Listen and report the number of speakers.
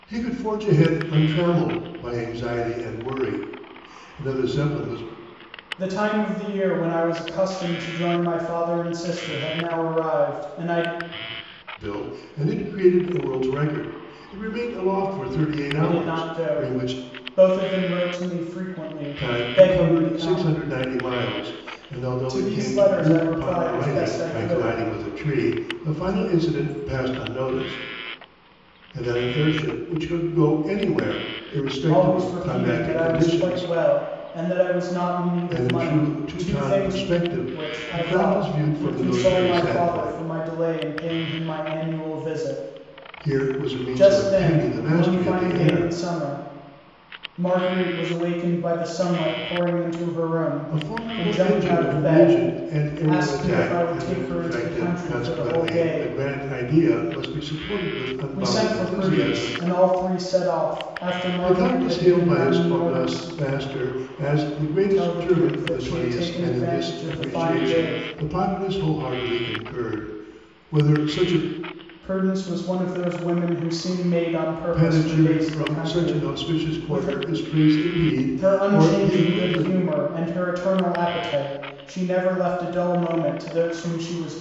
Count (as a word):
two